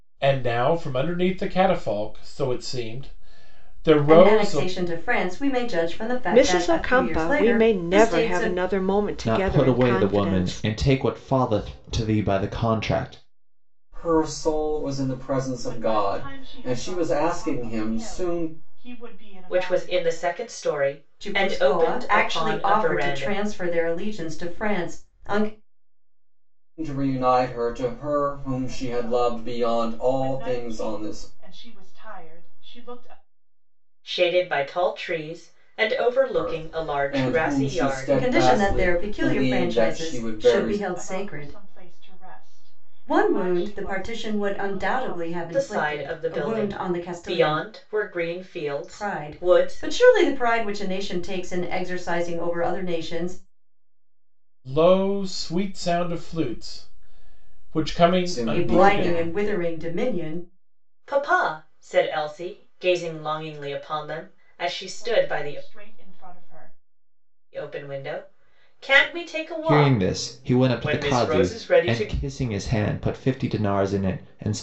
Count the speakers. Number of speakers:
7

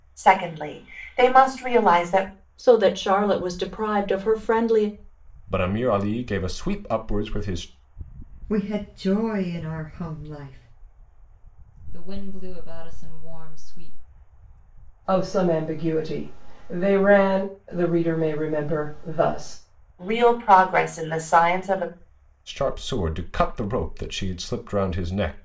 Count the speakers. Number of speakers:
6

